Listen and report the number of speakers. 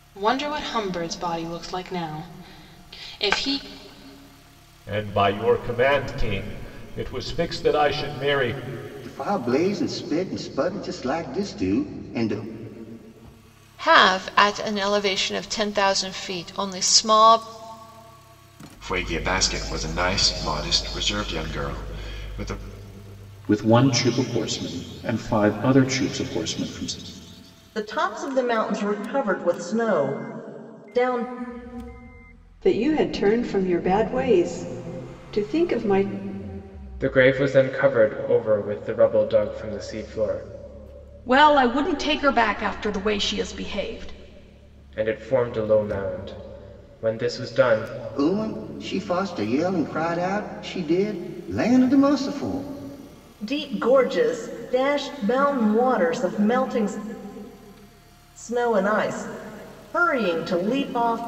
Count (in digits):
10